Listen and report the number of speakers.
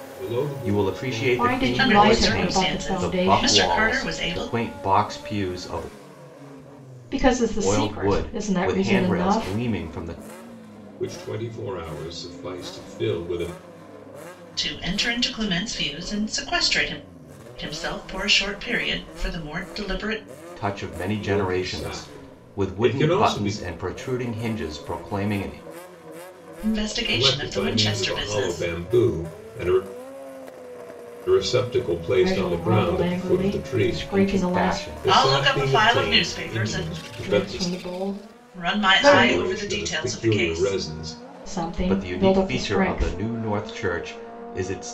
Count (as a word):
four